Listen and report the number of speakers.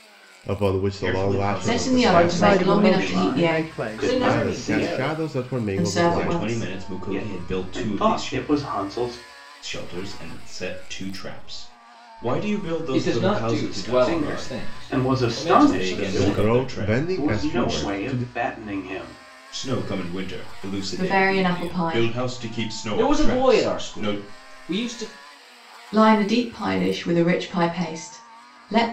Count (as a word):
six